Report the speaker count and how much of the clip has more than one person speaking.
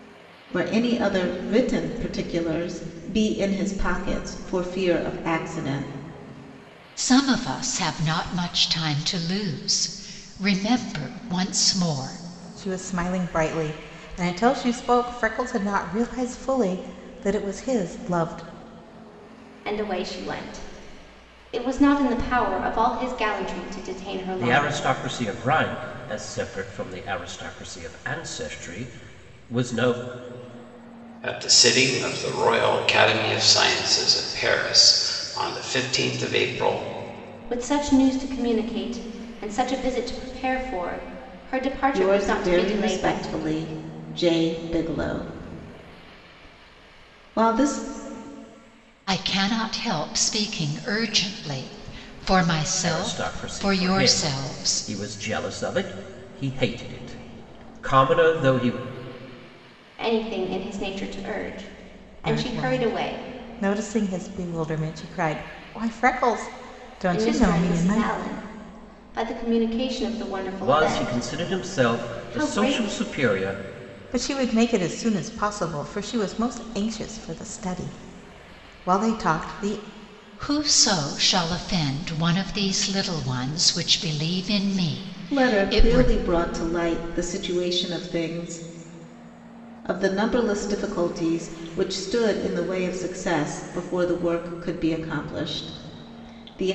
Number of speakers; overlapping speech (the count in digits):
6, about 10%